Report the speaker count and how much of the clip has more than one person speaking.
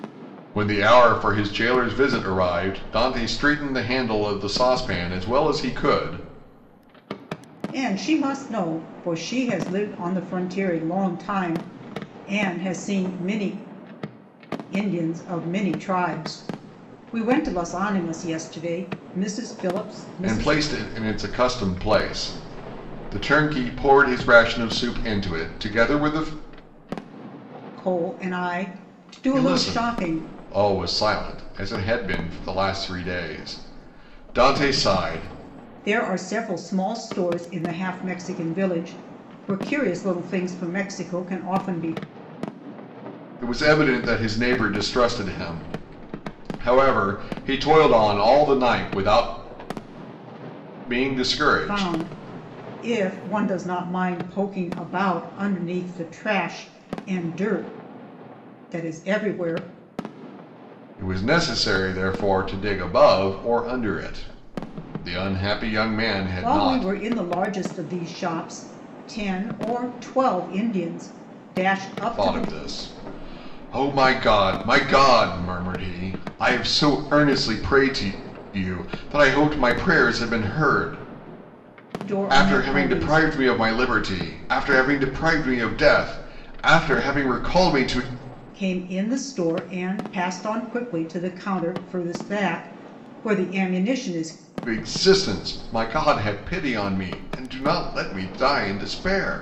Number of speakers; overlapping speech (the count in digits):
2, about 4%